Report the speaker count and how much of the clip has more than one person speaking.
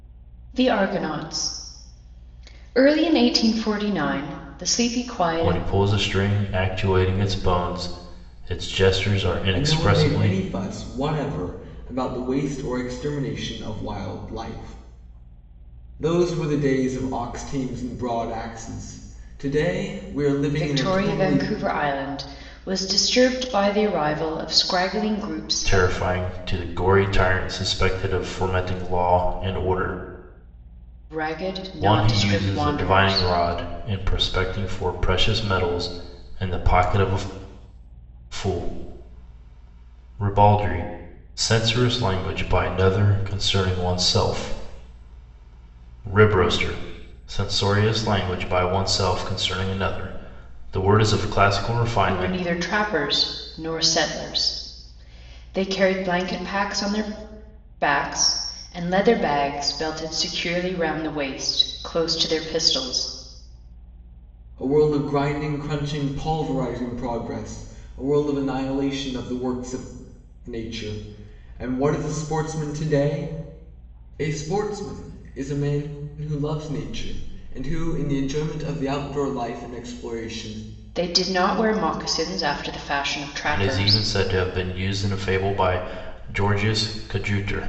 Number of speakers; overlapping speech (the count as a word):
three, about 6%